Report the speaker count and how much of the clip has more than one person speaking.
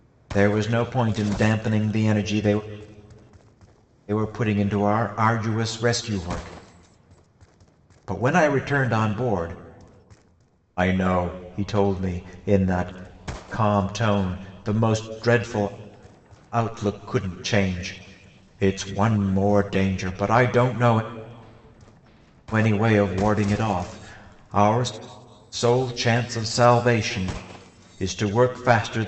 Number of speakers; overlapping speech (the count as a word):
one, no overlap